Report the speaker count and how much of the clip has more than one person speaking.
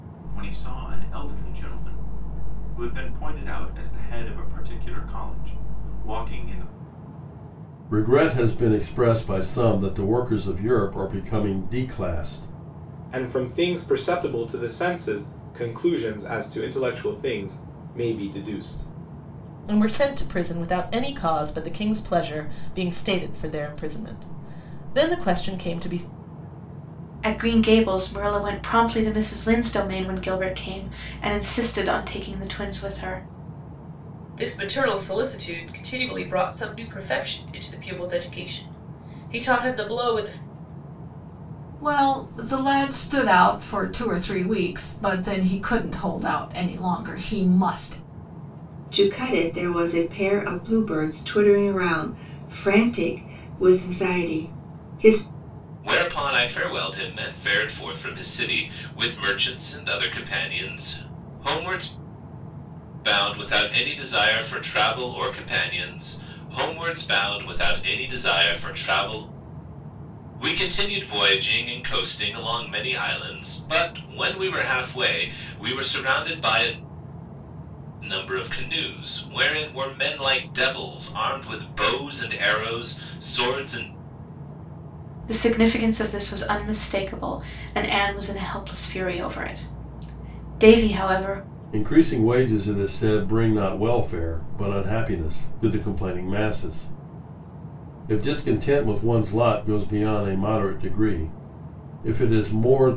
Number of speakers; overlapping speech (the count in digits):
9, no overlap